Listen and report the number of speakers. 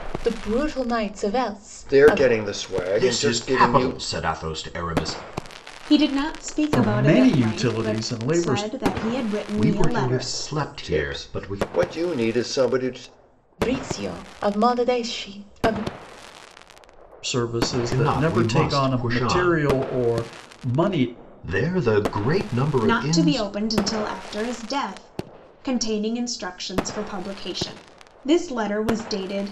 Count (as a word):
five